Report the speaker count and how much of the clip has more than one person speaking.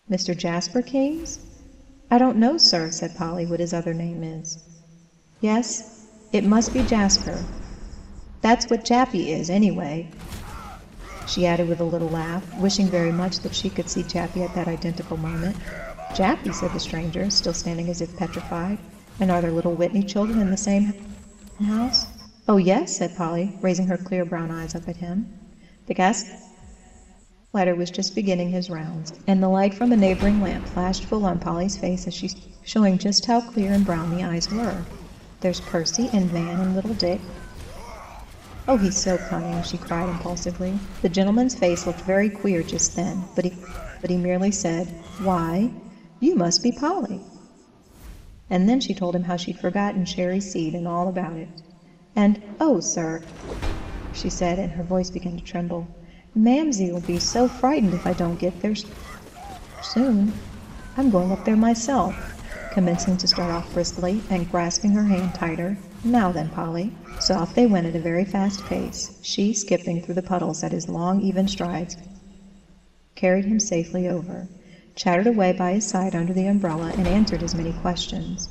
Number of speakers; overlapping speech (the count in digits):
1, no overlap